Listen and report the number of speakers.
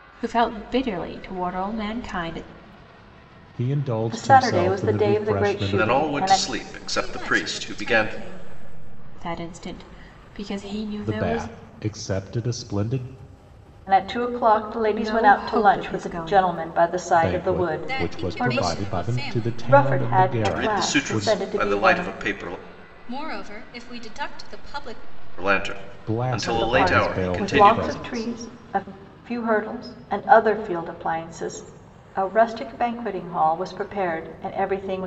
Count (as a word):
five